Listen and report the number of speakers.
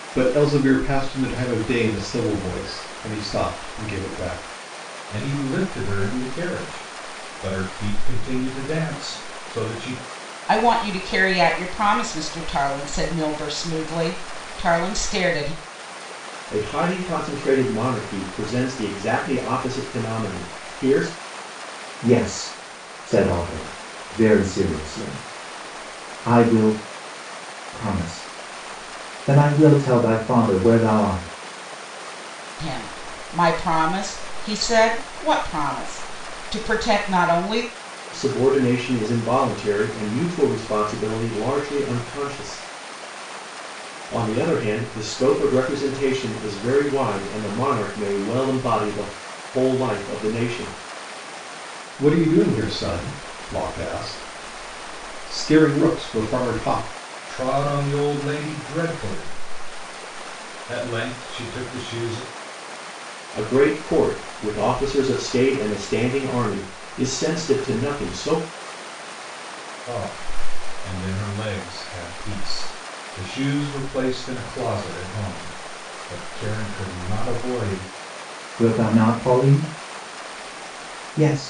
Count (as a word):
five